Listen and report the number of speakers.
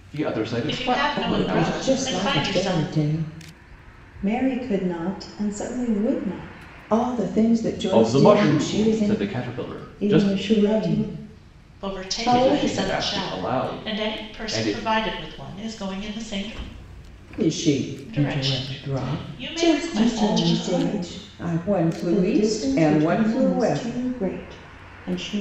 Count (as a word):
four